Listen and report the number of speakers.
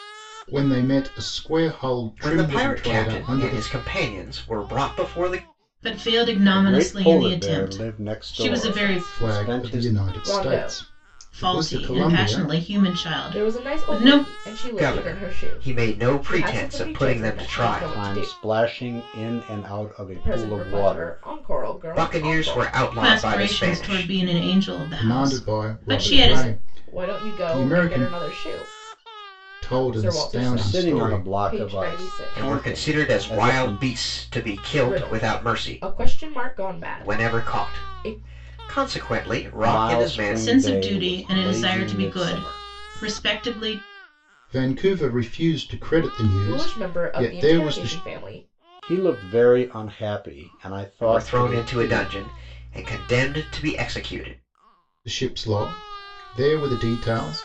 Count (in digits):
5